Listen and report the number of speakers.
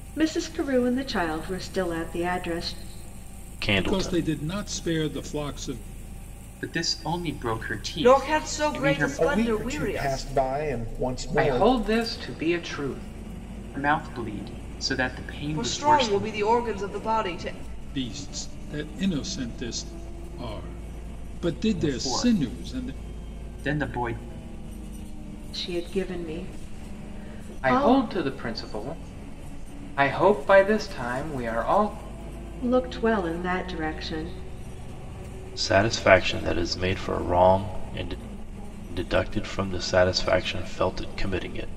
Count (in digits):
7